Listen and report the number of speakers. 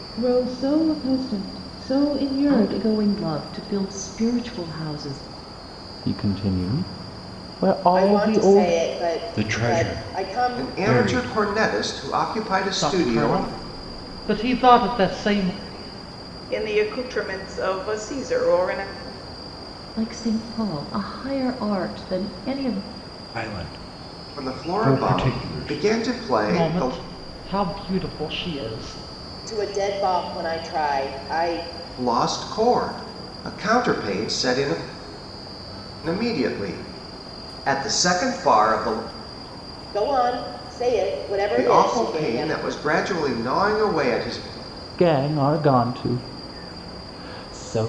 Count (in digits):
8